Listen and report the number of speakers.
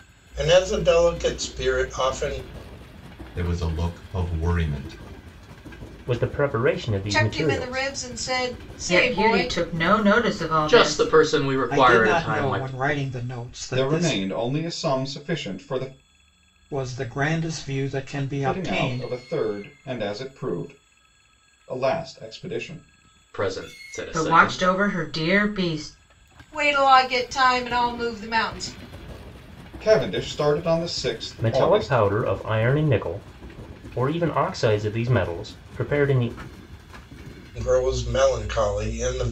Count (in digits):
8